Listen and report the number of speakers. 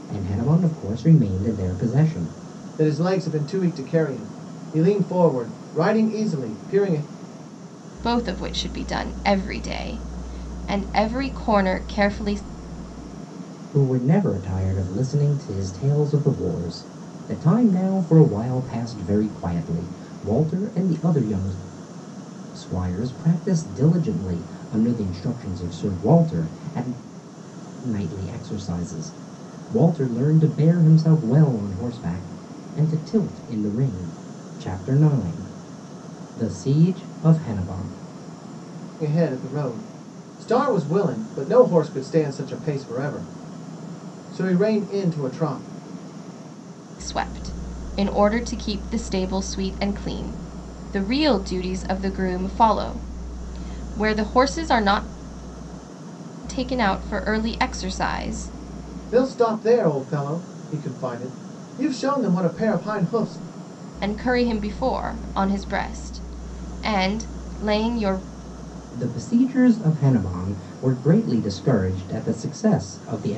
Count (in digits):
3